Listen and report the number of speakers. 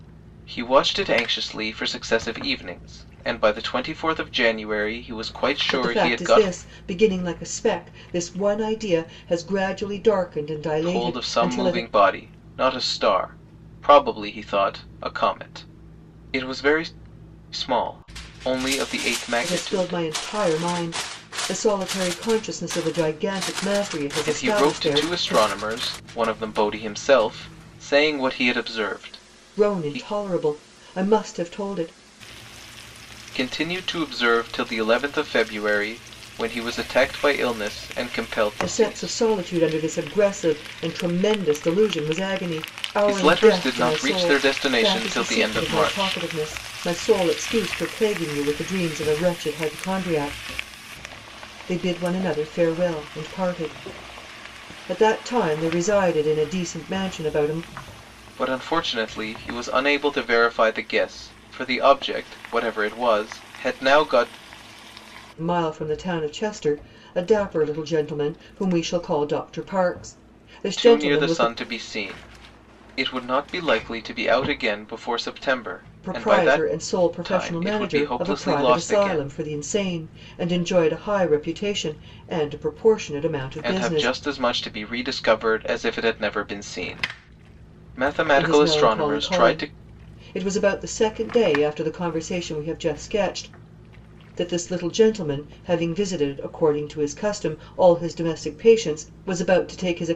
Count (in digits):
2